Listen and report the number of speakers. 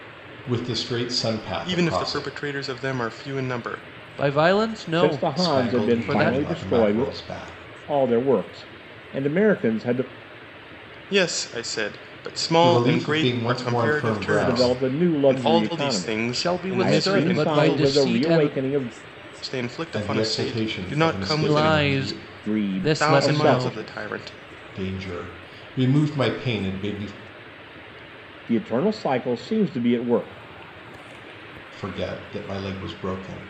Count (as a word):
four